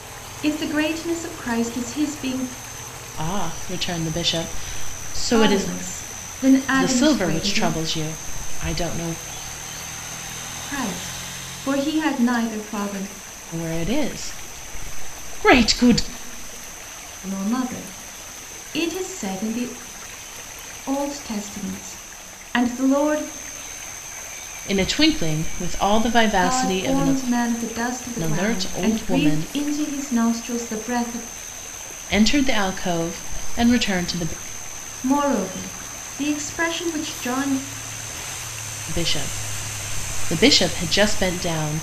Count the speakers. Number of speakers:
2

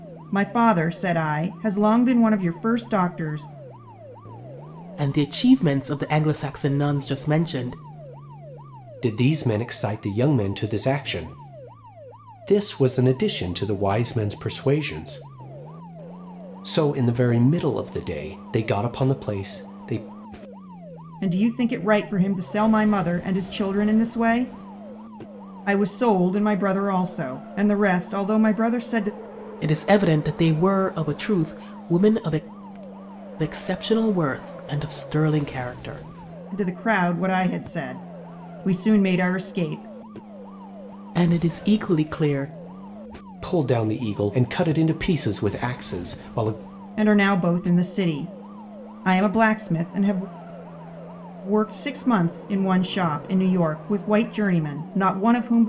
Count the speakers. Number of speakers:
3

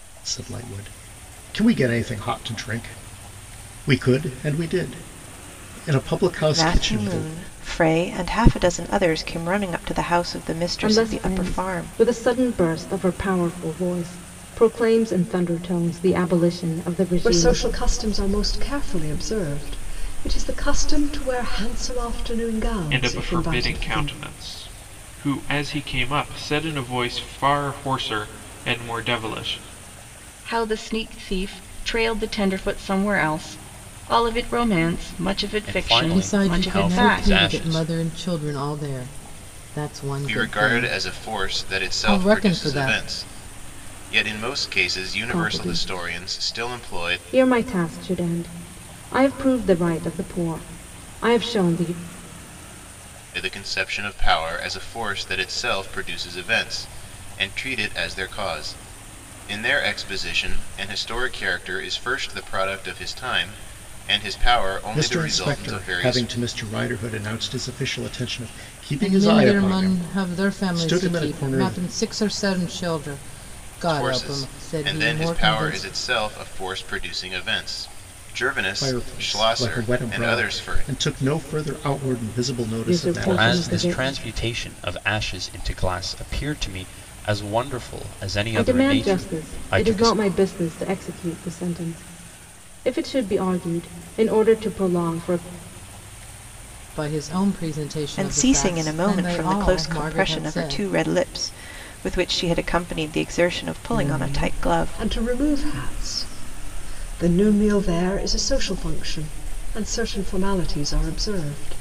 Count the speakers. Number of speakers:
9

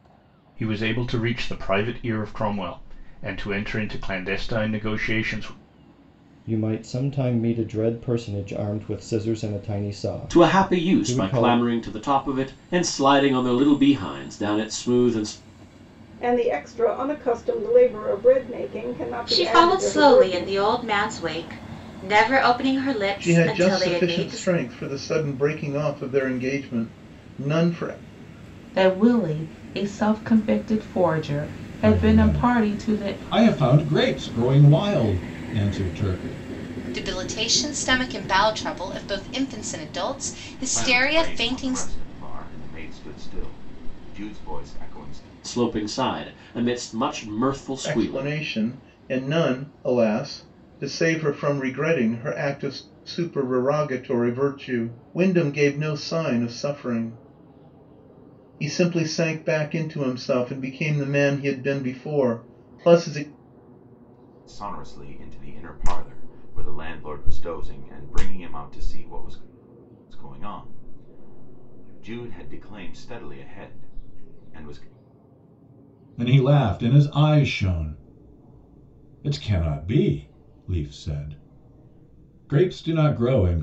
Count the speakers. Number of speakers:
10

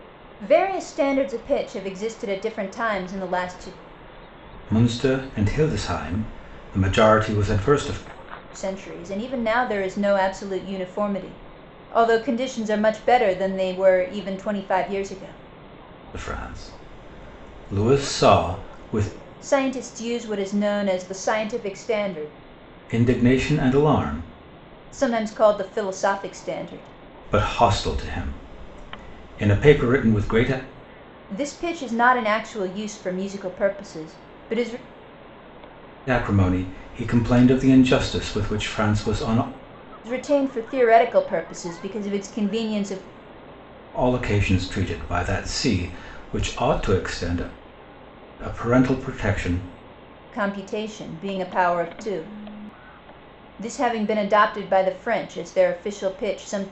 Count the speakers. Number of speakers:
2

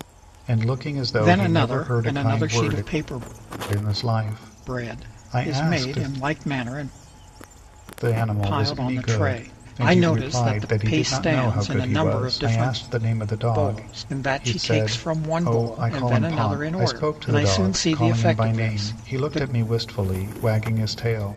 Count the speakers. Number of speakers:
2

